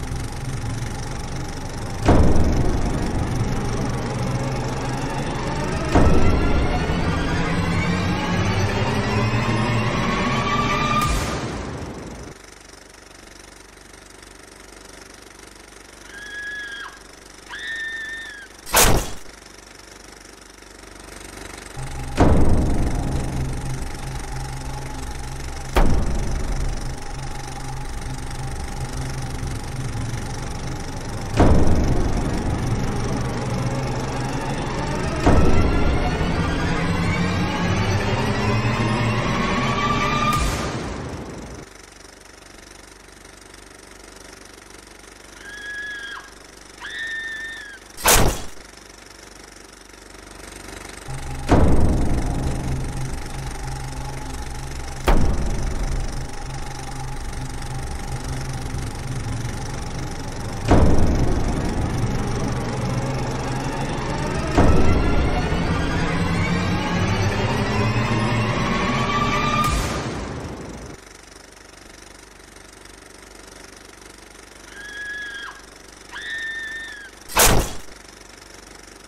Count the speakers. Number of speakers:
zero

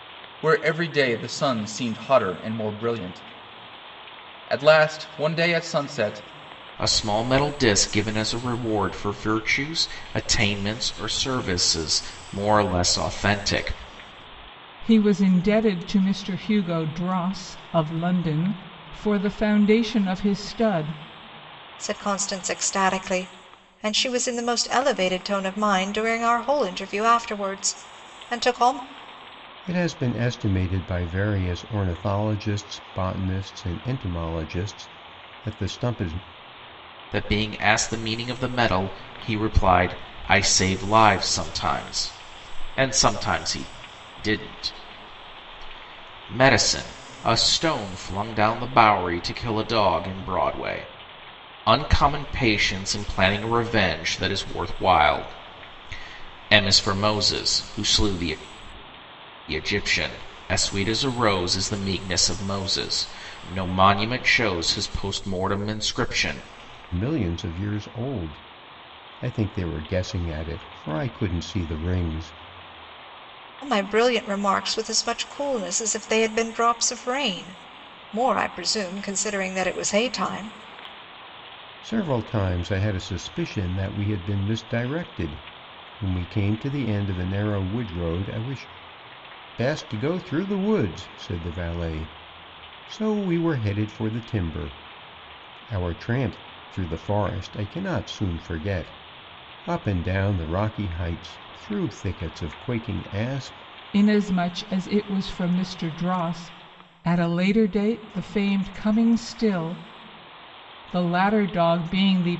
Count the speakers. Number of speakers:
five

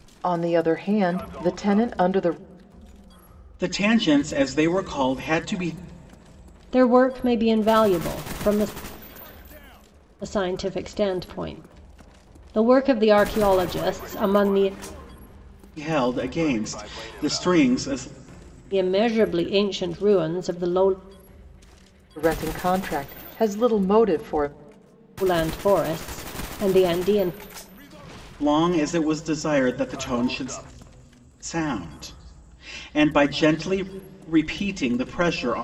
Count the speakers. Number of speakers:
three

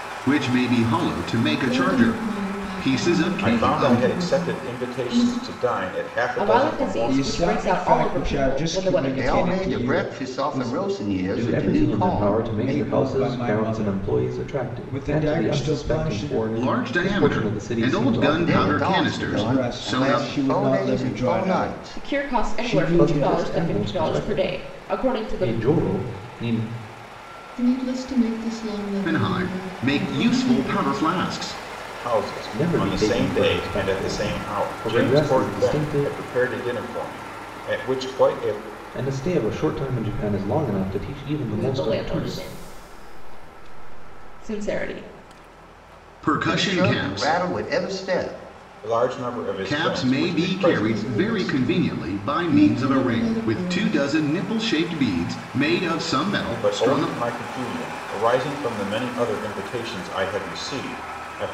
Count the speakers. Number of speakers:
seven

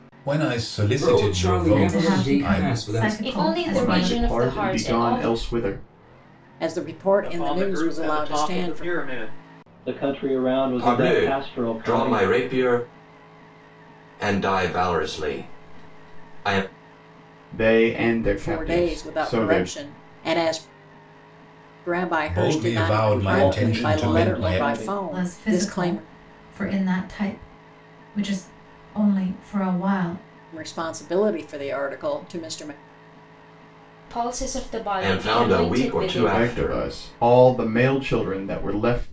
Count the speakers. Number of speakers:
nine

